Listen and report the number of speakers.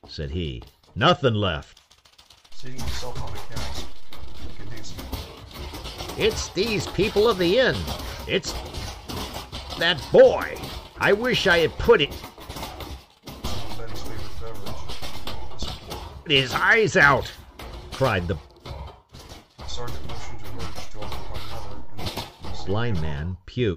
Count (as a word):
two